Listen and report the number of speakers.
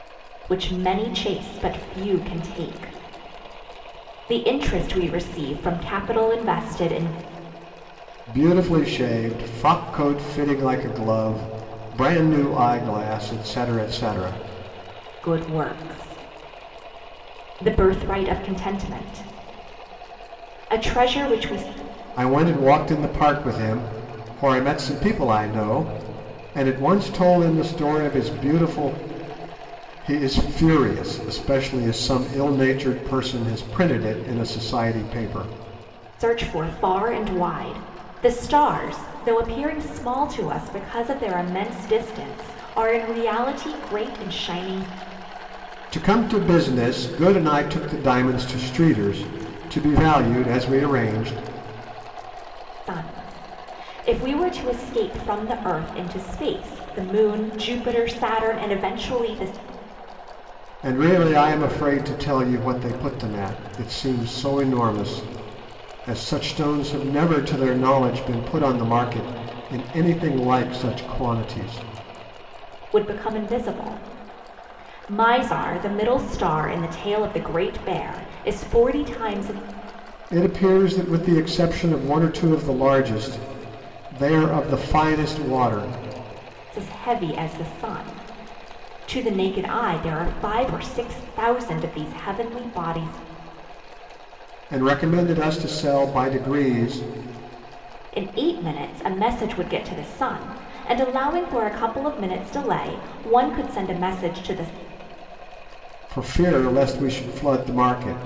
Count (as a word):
two